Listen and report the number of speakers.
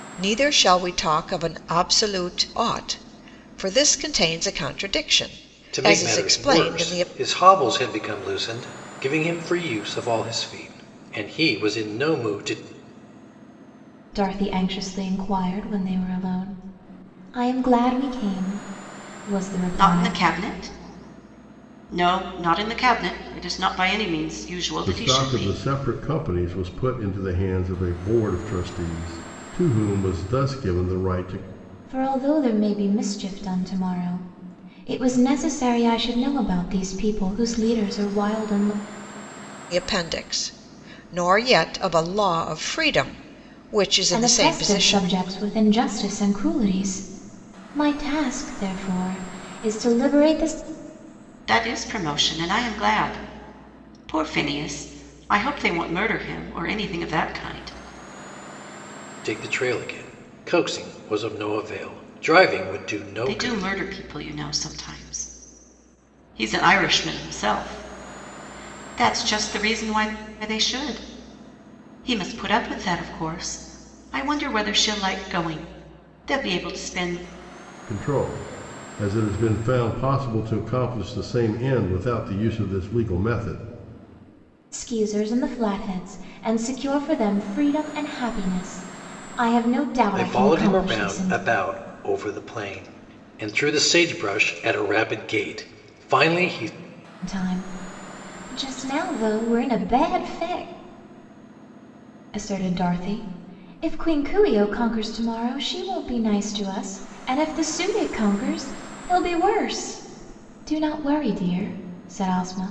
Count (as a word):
five